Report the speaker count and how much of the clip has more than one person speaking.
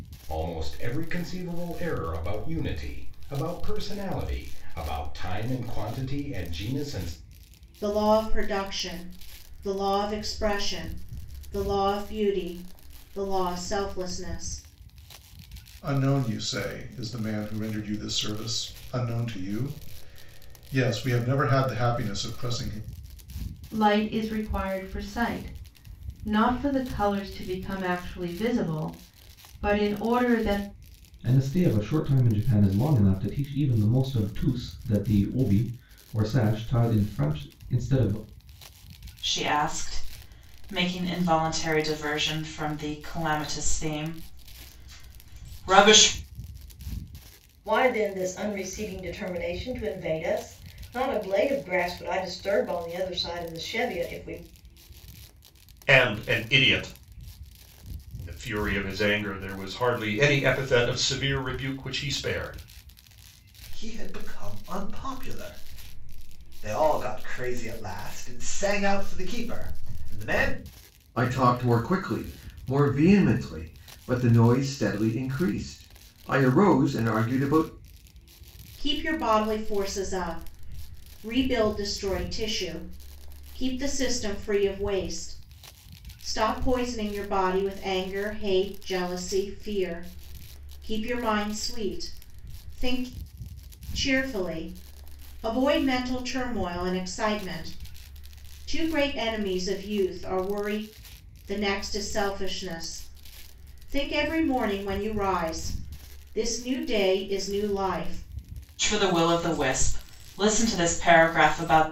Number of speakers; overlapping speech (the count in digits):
10, no overlap